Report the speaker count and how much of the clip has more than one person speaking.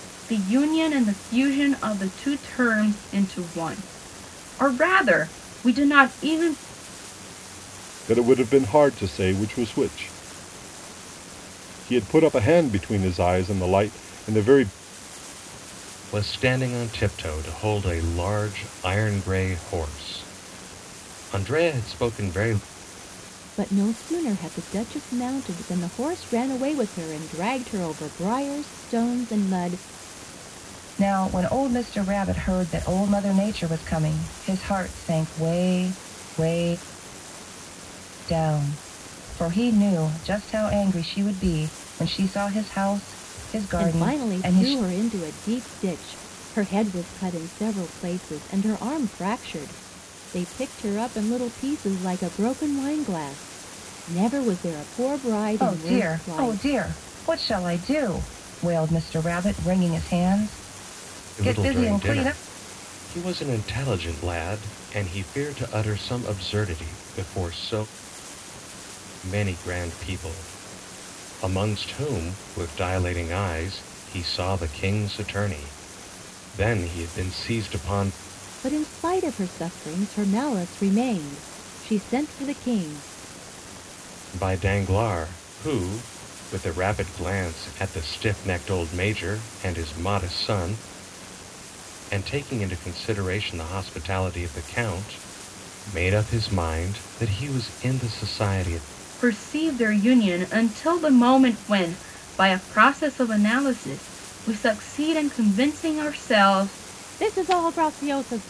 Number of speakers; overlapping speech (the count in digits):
5, about 3%